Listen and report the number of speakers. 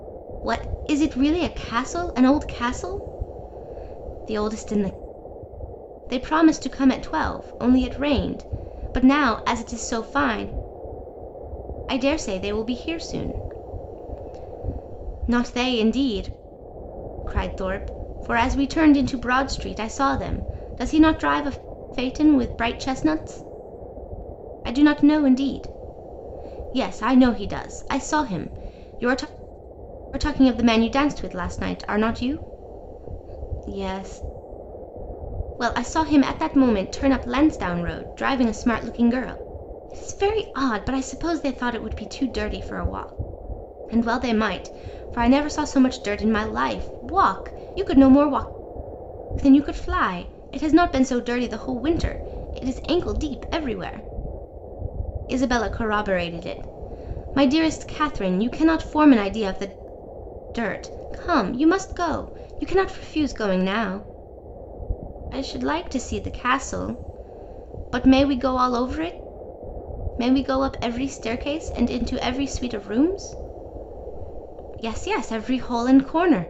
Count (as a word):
one